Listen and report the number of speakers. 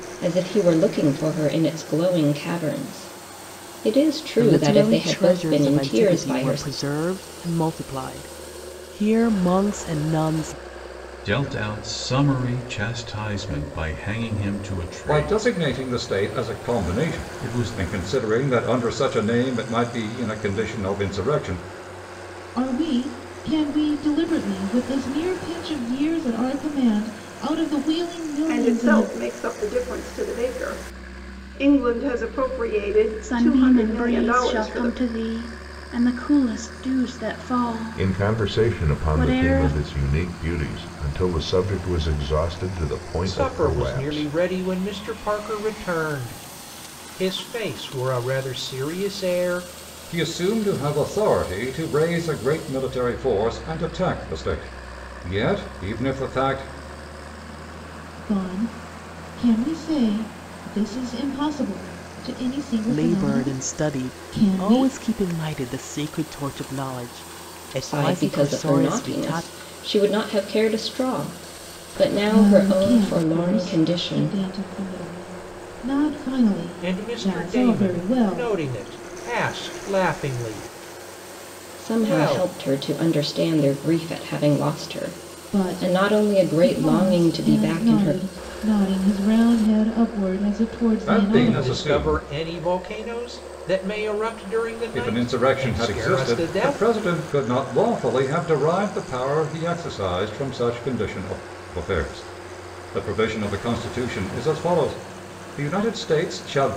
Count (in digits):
9